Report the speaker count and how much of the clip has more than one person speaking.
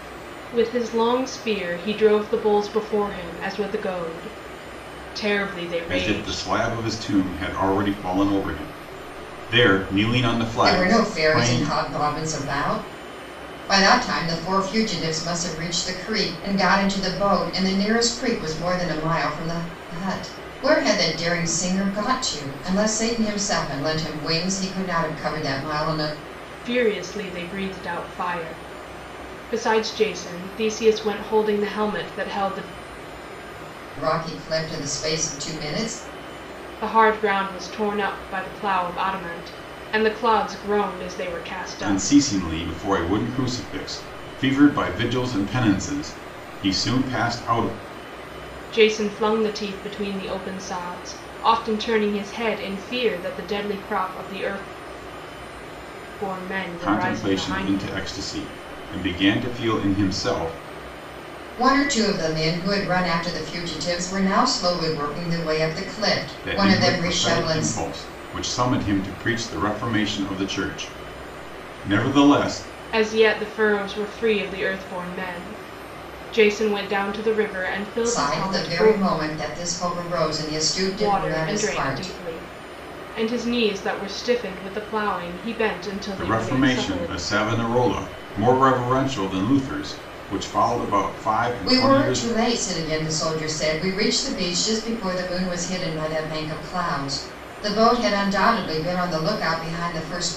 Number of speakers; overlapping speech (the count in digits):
3, about 9%